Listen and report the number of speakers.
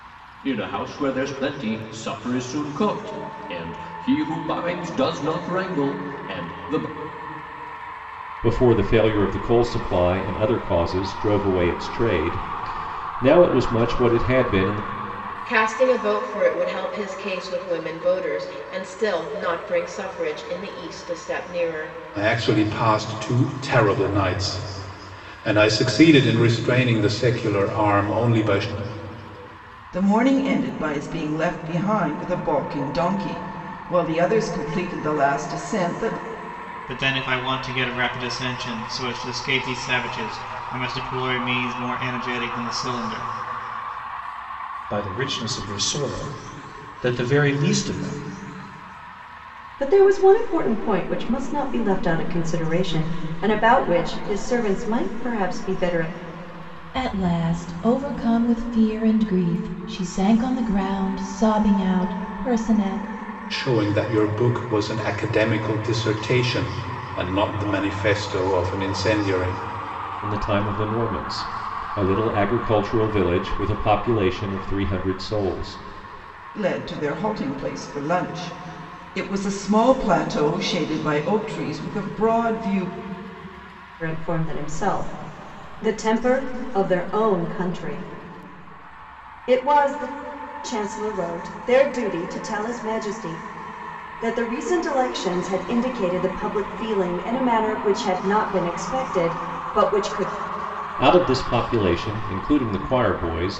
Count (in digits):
9